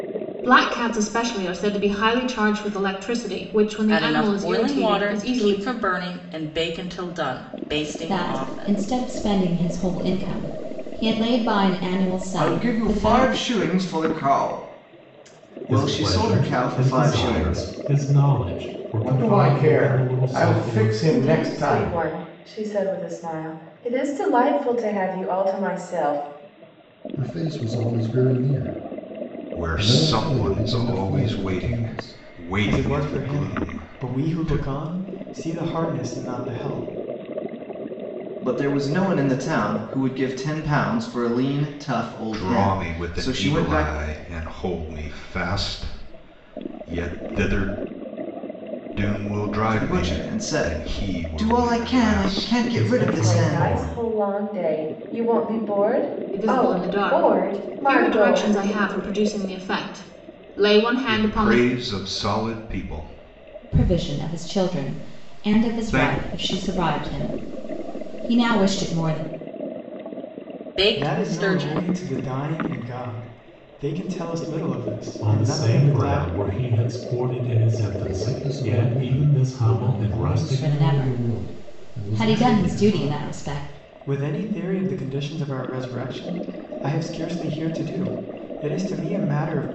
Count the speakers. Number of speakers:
10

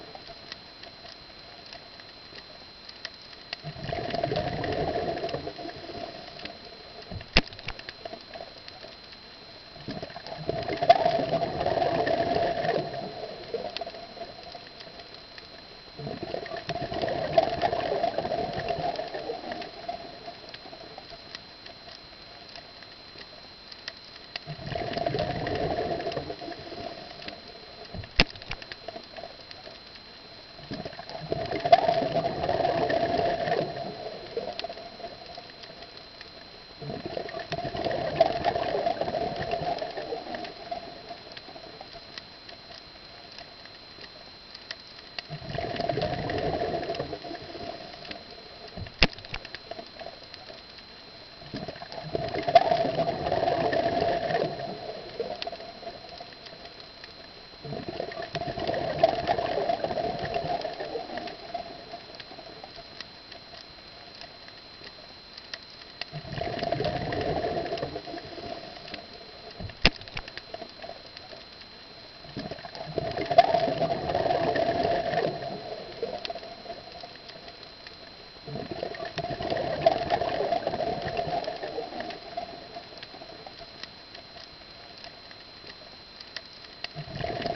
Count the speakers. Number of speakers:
0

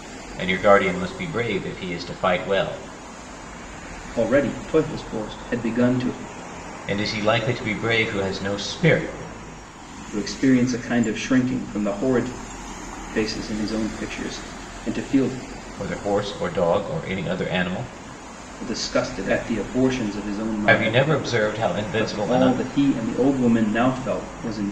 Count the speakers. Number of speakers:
2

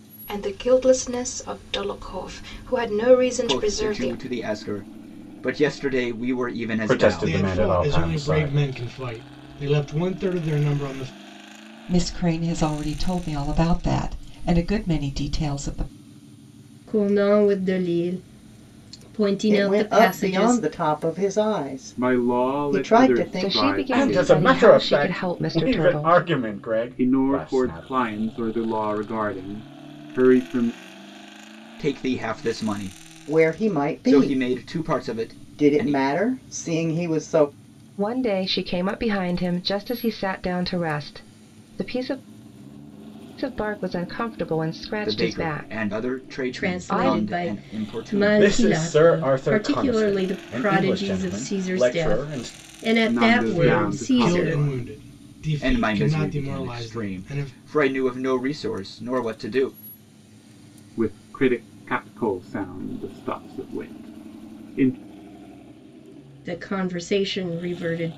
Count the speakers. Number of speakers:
9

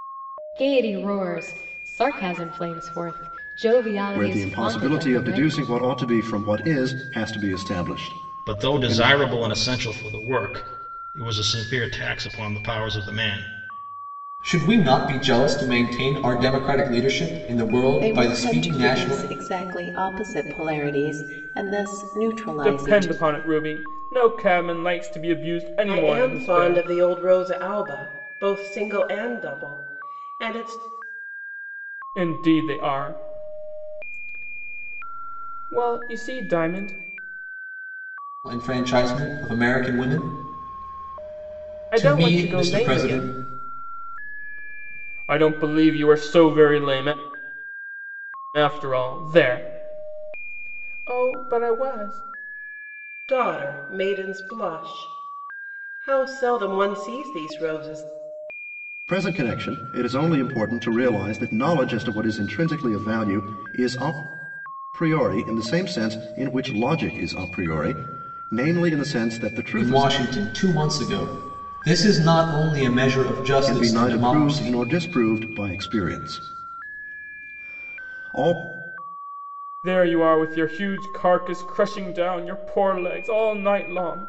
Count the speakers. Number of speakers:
7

